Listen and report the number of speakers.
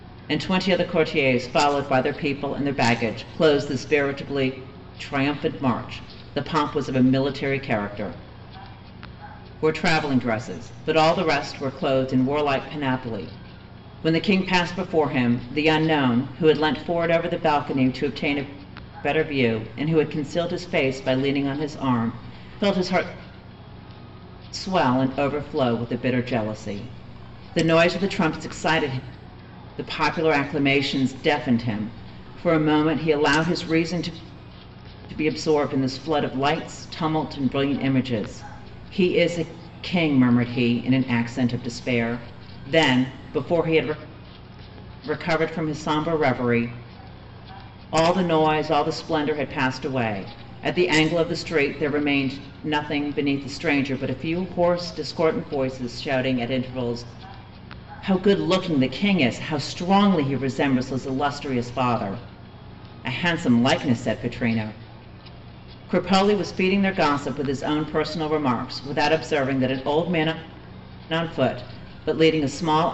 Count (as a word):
one